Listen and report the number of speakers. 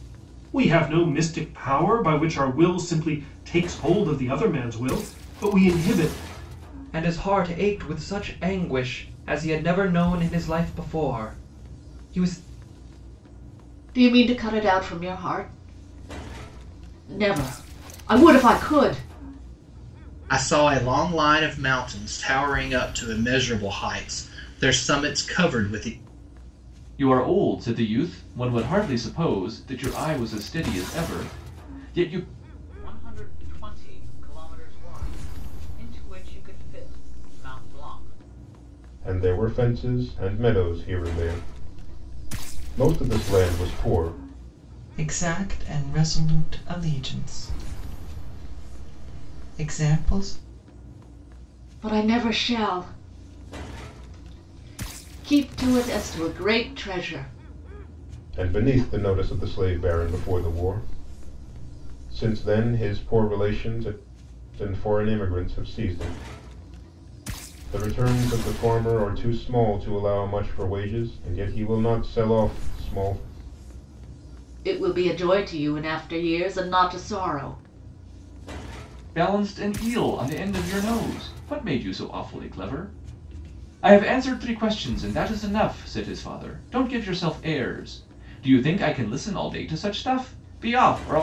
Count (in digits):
8